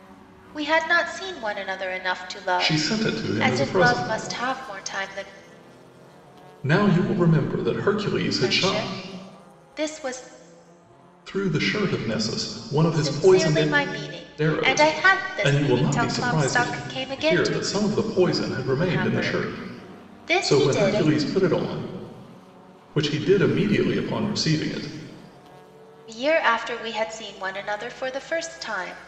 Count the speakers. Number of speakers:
two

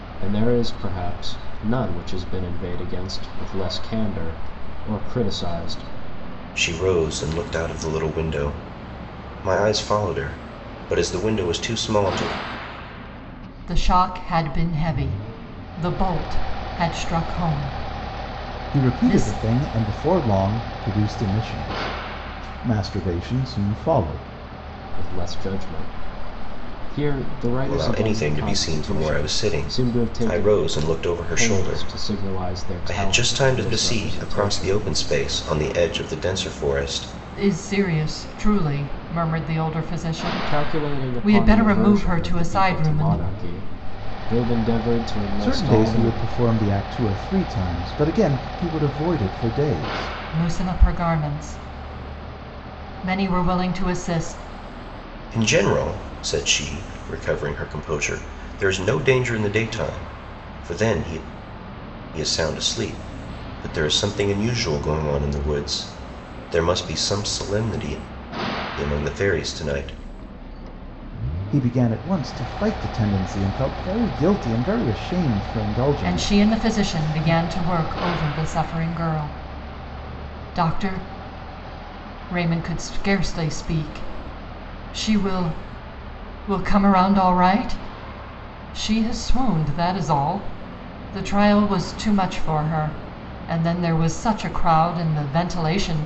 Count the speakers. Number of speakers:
four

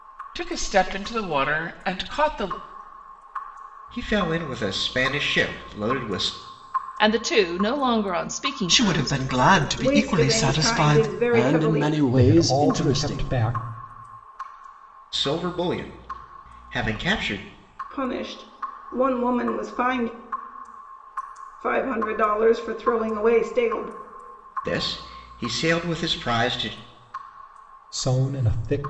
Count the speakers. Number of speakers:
seven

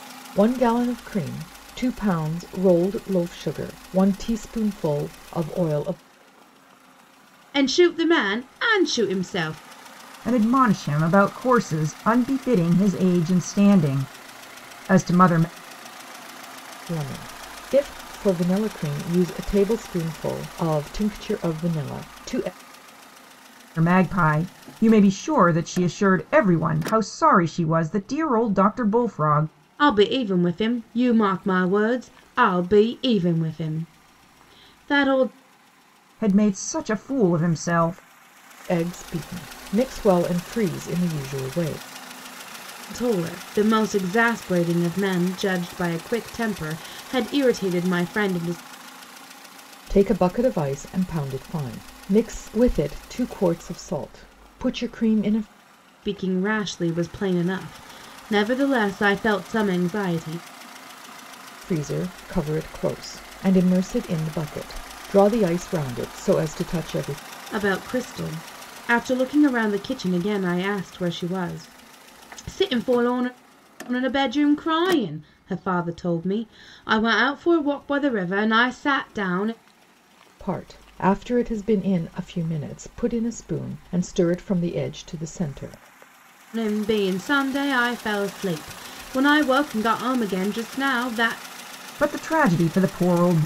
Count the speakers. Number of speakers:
three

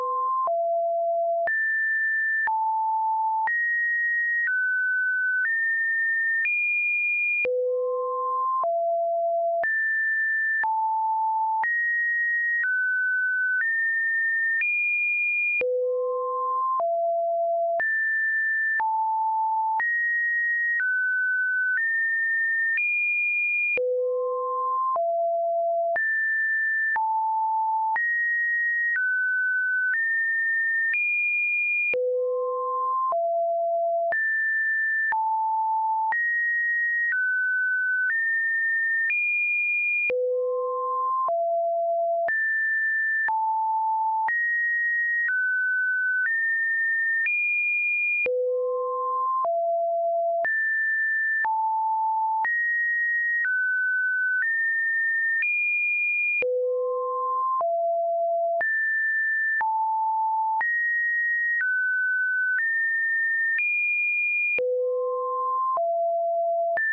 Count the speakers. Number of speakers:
zero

